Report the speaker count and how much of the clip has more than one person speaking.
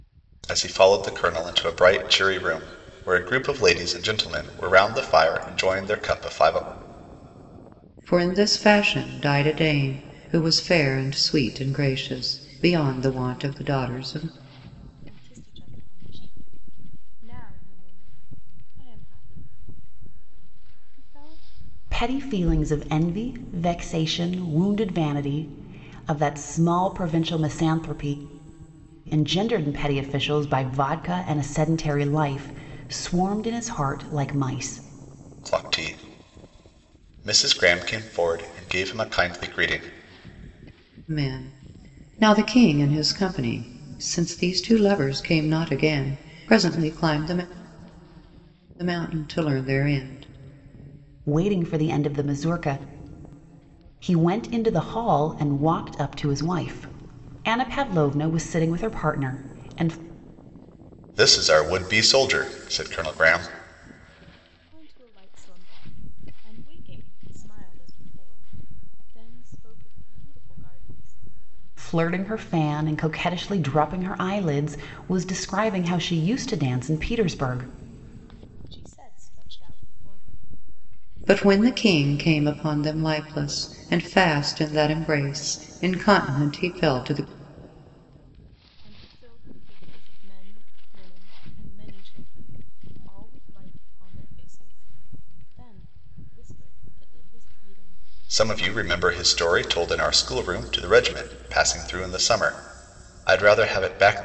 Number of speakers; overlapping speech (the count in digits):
4, no overlap